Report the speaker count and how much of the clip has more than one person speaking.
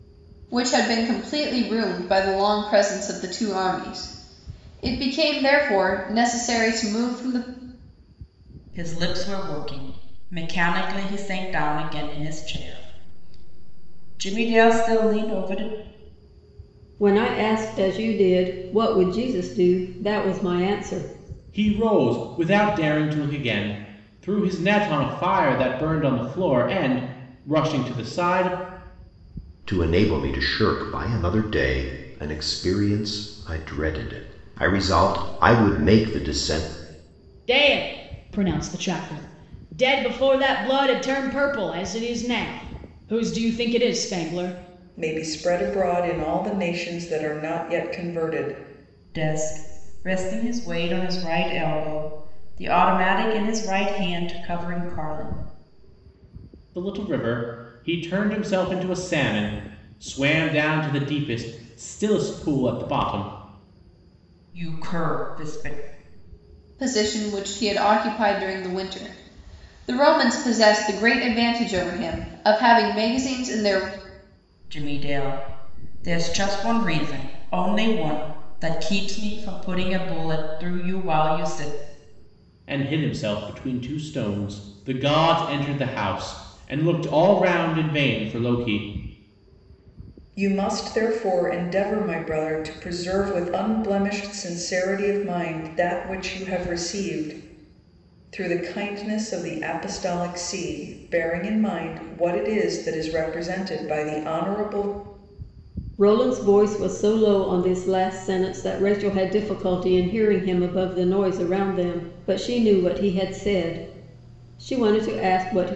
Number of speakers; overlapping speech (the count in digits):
7, no overlap